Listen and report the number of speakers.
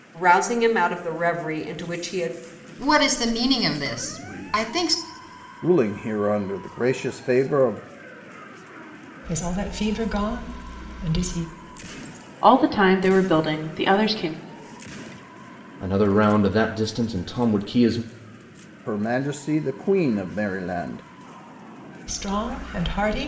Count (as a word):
six